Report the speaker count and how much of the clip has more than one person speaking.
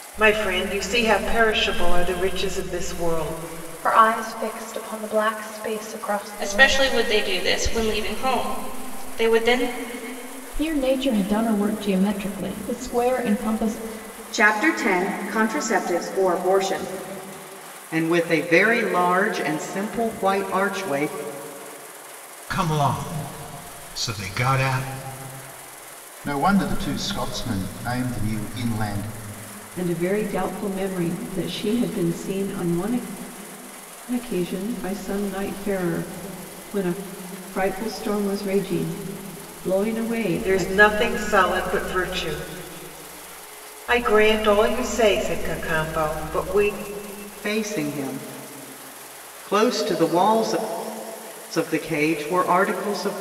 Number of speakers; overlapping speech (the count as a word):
nine, about 2%